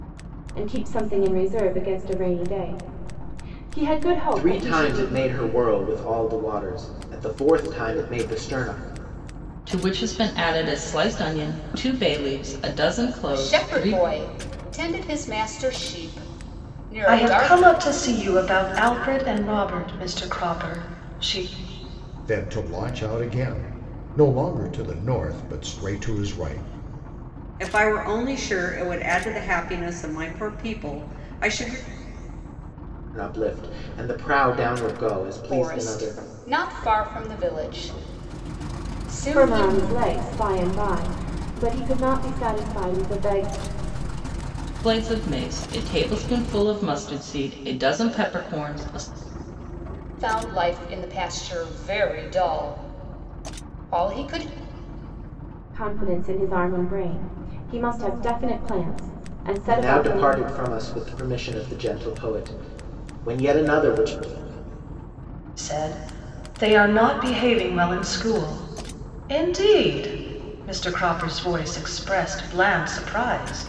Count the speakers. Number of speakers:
7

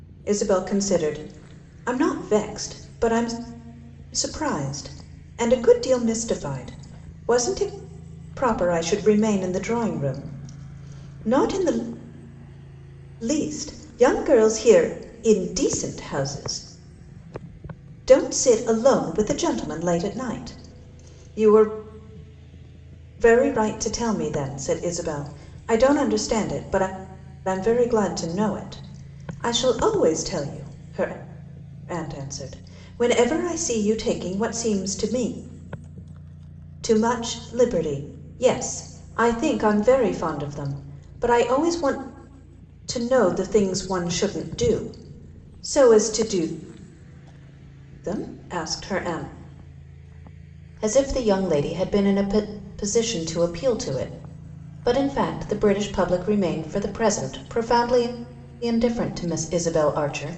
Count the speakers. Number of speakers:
1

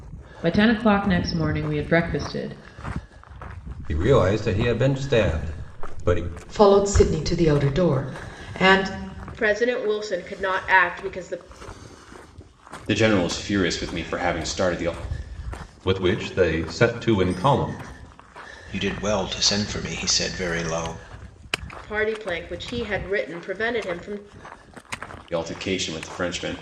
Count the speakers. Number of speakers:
7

